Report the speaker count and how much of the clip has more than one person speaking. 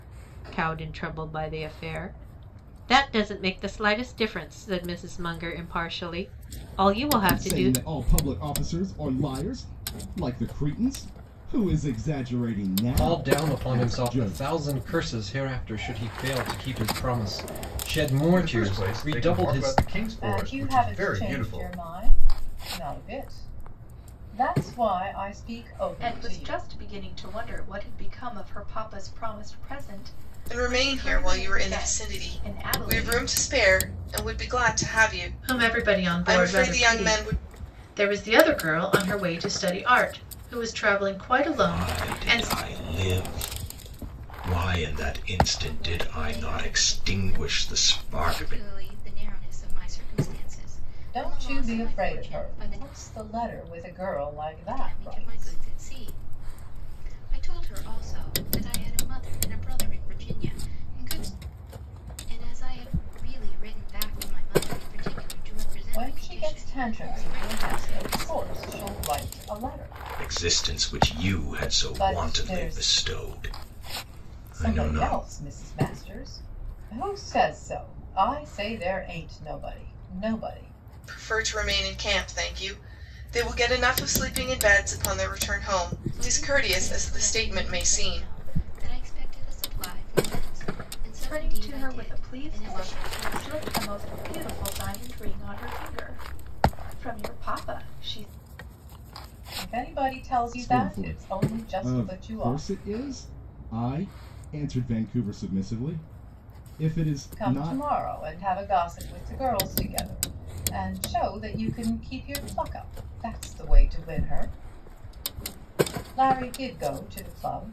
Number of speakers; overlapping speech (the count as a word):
ten, about 26%